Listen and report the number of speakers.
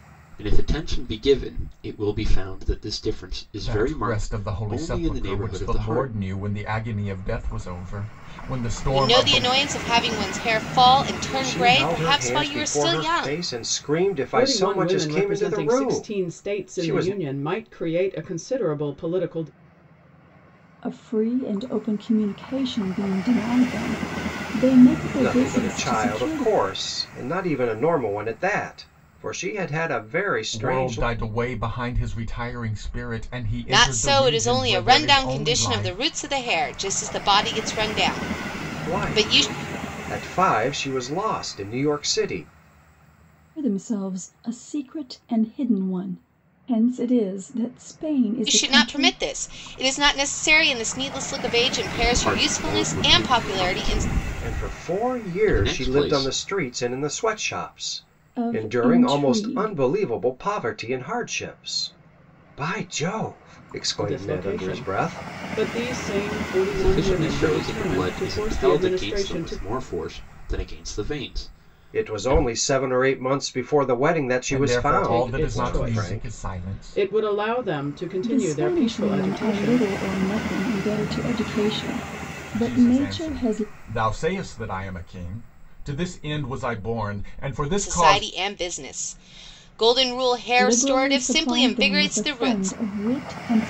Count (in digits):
6